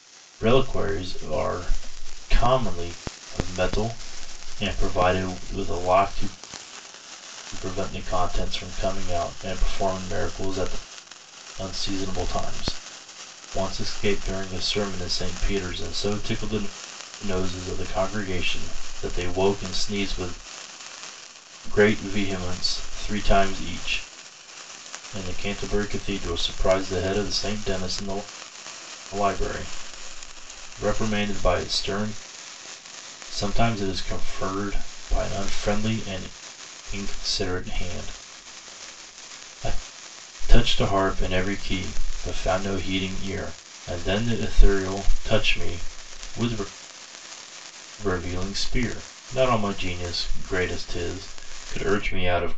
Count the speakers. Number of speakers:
1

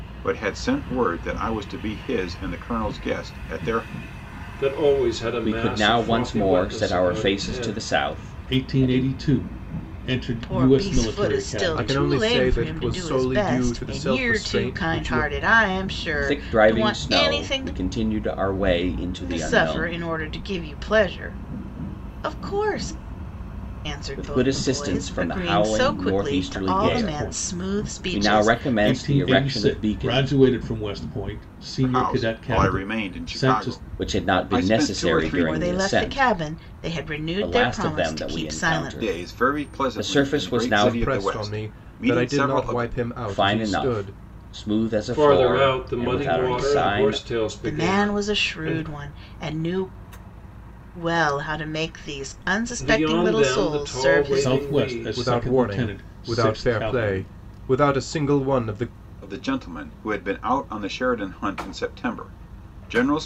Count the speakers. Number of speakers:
6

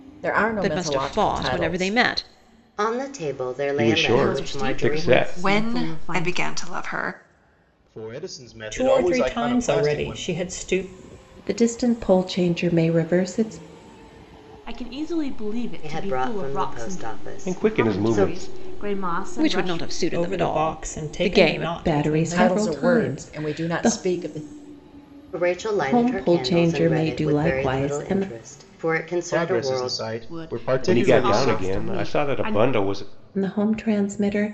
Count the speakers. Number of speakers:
9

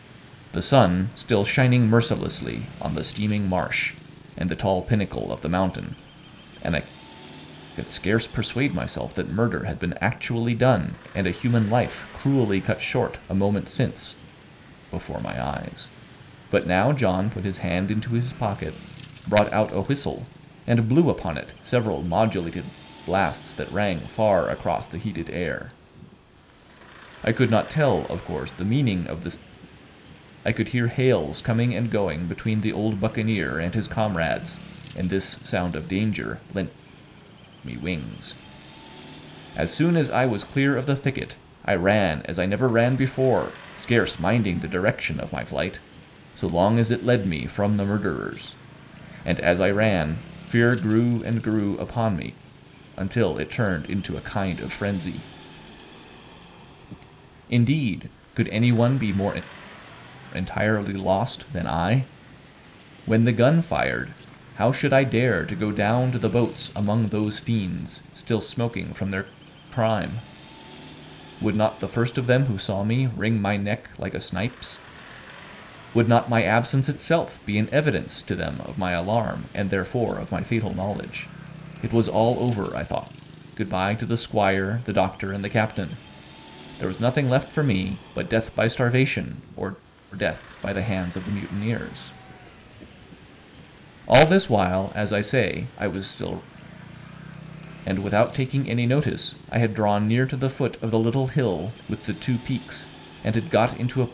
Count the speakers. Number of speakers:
1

